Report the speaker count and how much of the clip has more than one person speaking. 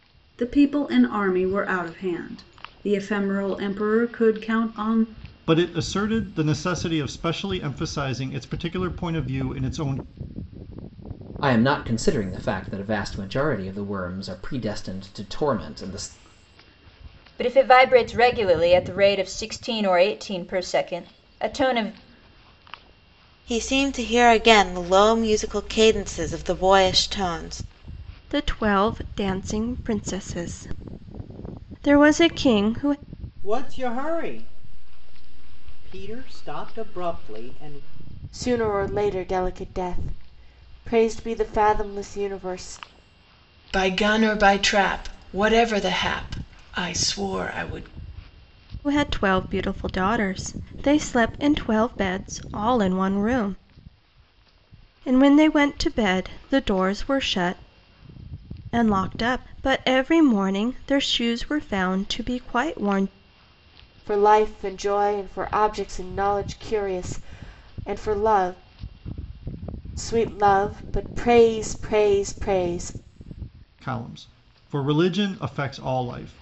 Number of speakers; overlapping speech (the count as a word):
nine, no overlap